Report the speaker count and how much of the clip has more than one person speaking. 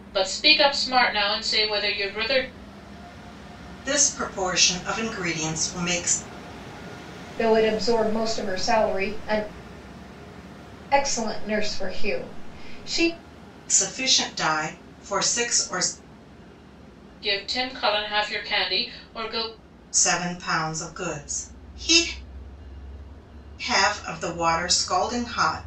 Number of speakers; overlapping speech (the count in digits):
3, no overlap